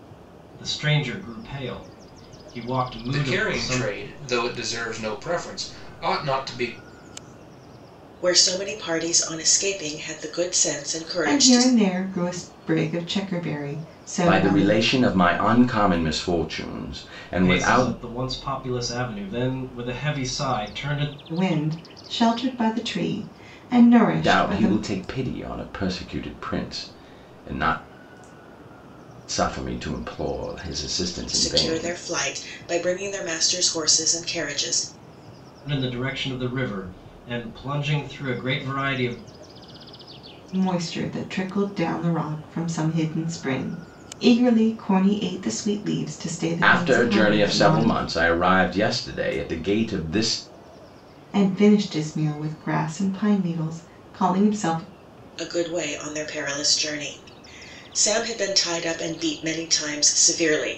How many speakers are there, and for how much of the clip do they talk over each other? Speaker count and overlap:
5, about 8%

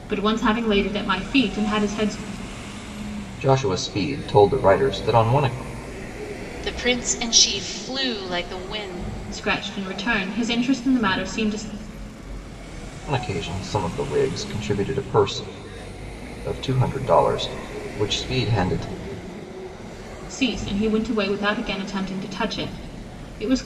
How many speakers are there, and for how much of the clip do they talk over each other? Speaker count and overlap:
3, no overlap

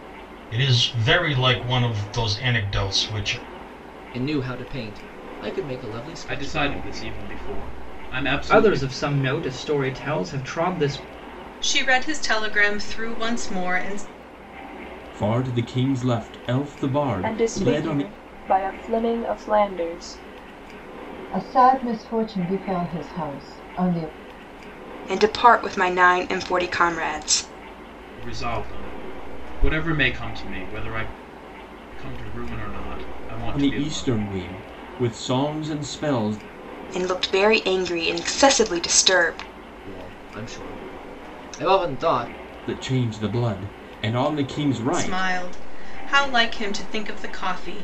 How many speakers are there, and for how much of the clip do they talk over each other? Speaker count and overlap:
9, about 6%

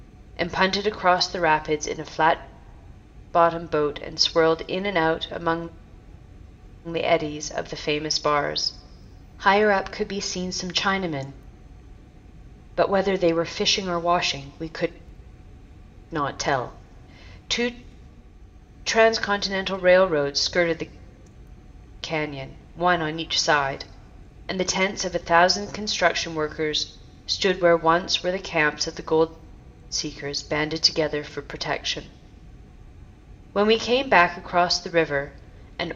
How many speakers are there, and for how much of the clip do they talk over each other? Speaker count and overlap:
1, no overlap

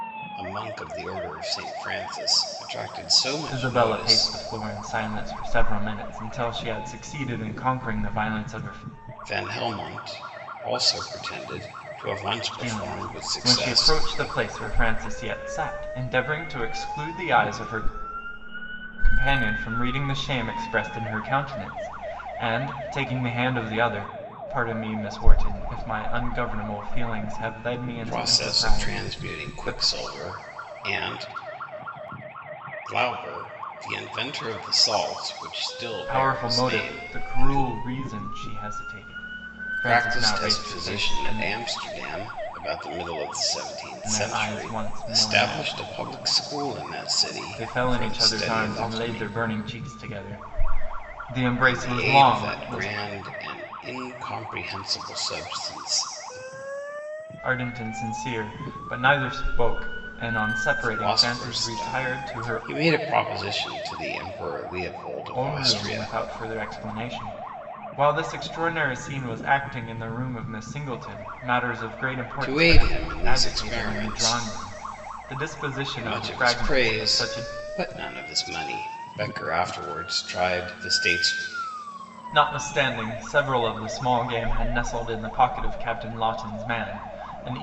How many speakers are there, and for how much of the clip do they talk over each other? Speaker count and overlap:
2, about 21%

